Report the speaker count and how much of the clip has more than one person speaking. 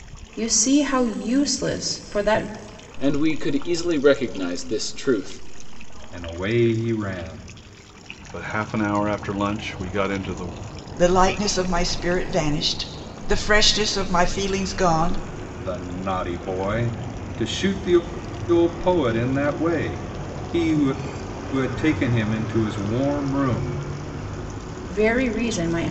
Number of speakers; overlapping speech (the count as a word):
five, no overlap